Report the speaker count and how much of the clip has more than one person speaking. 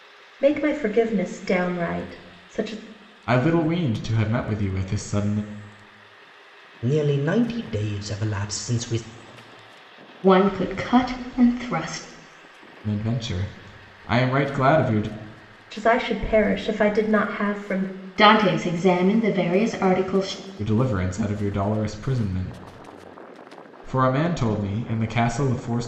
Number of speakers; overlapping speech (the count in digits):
4, no overlap